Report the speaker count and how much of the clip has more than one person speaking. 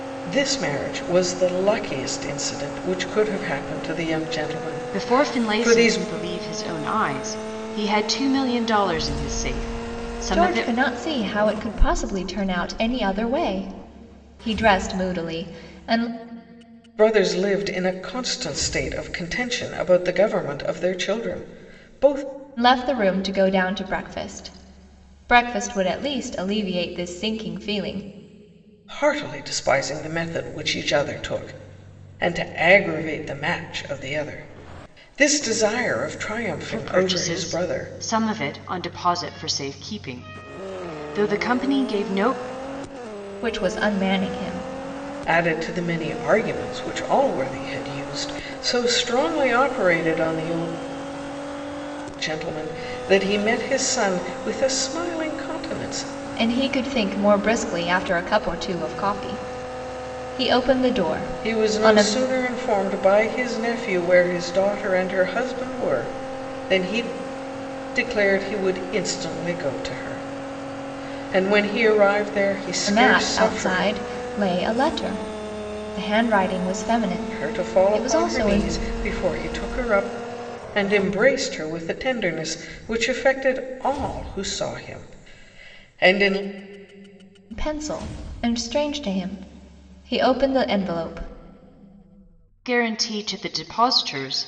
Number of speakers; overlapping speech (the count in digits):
3, about 6%